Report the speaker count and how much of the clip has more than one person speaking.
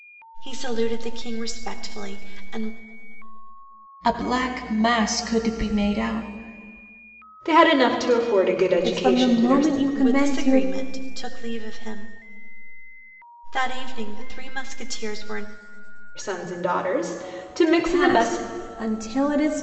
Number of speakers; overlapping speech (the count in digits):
4, about 12%